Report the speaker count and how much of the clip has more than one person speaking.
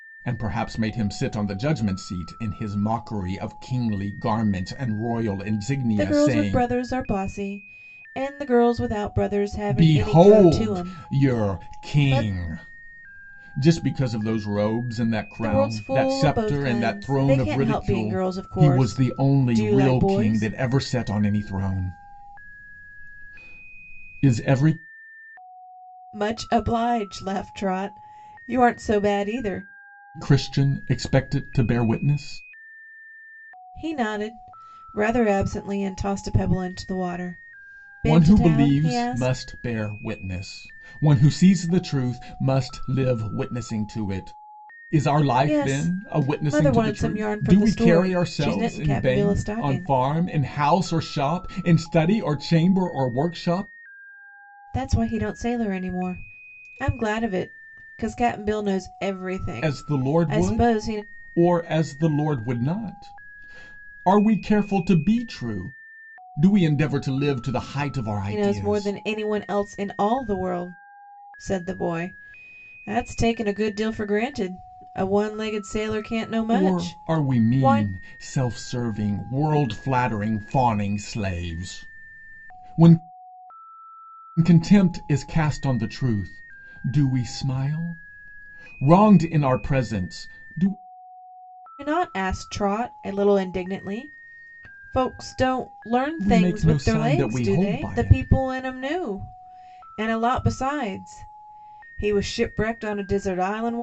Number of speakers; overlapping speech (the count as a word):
two, about 19%